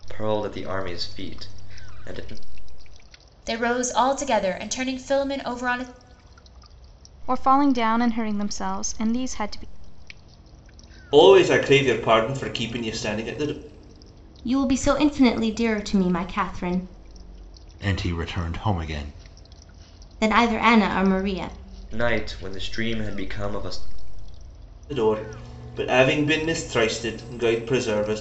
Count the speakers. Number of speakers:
six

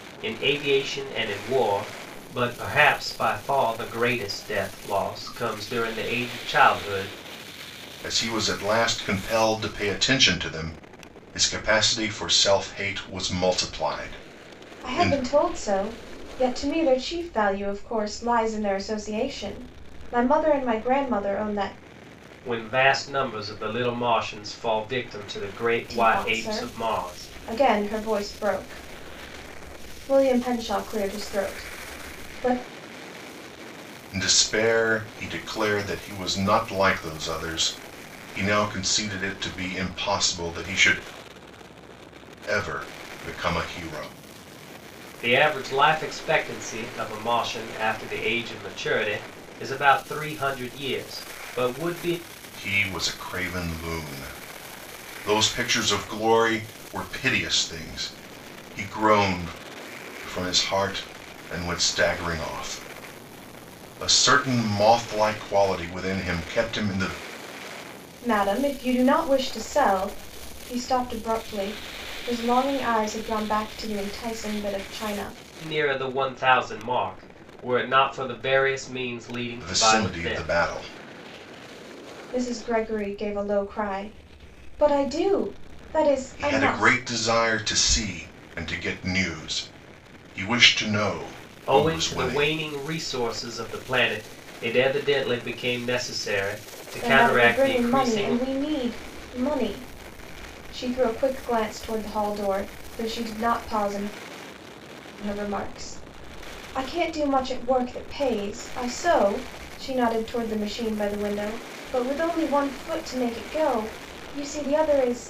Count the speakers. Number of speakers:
three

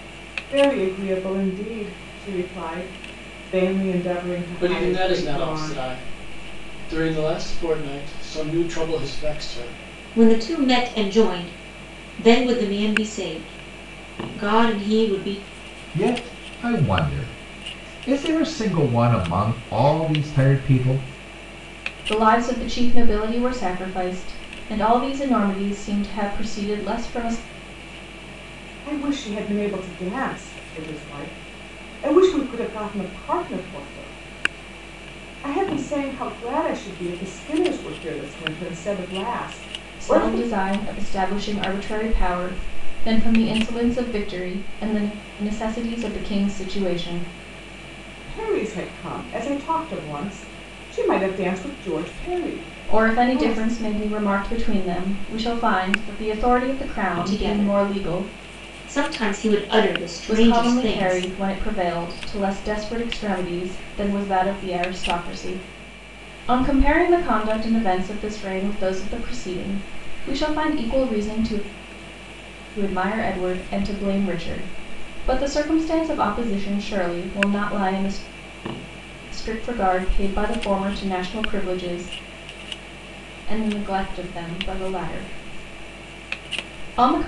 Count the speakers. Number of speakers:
five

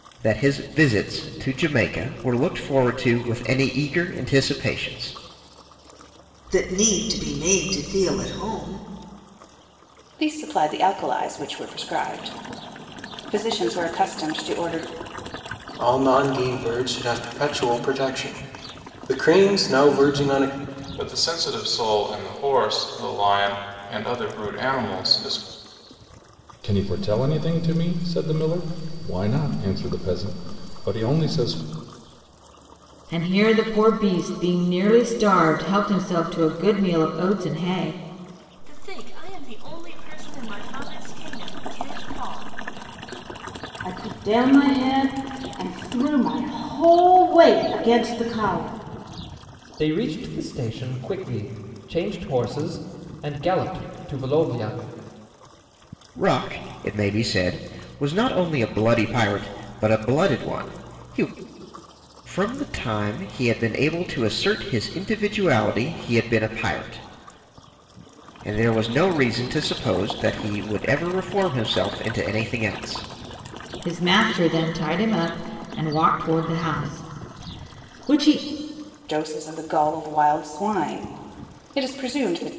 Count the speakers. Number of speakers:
ten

